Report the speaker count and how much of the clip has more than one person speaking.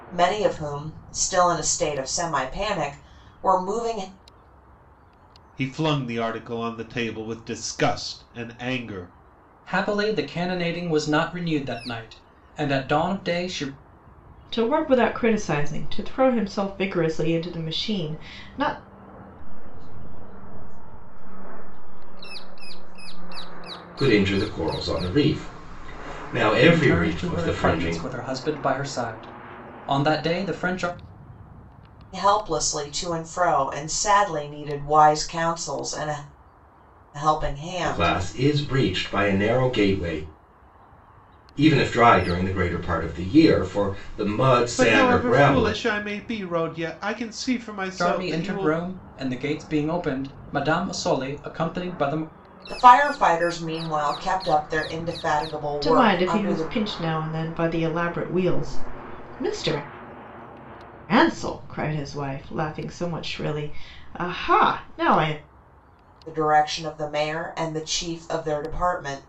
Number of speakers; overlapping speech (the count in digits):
6, about 7%